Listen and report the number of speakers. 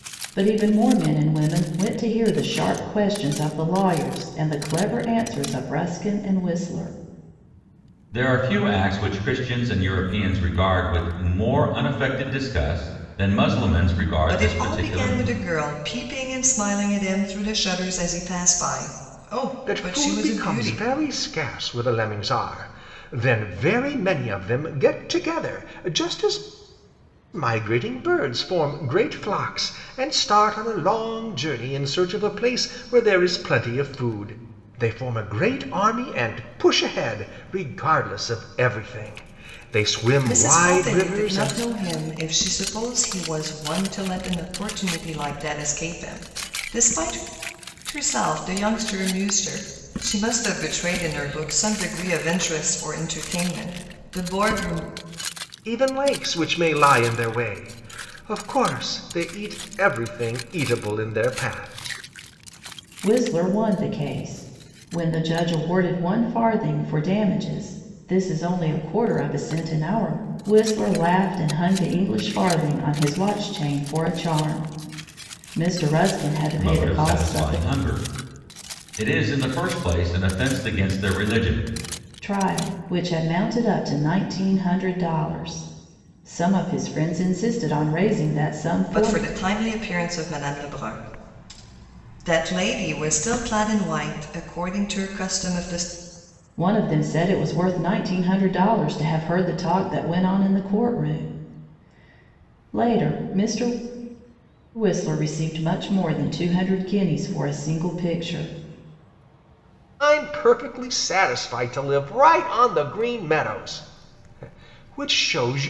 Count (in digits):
4